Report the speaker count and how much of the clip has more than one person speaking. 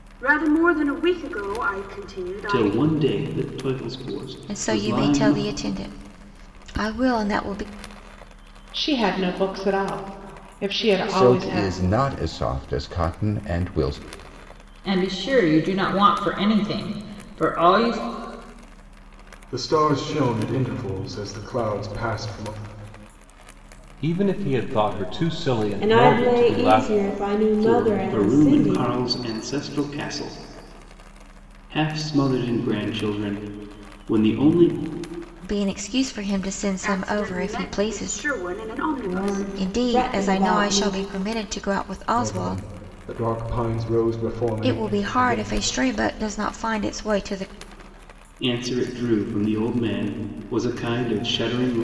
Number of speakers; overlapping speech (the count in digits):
9, about 18%